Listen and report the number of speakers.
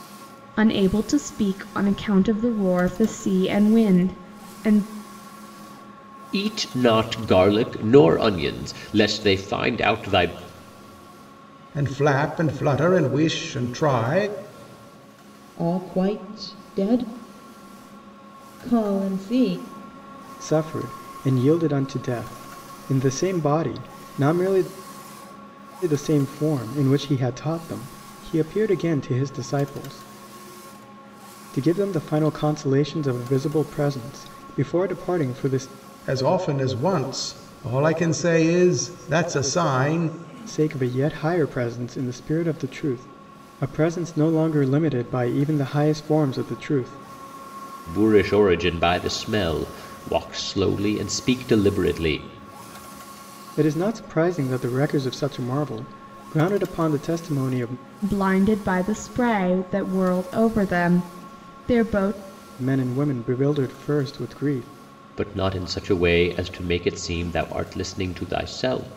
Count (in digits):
5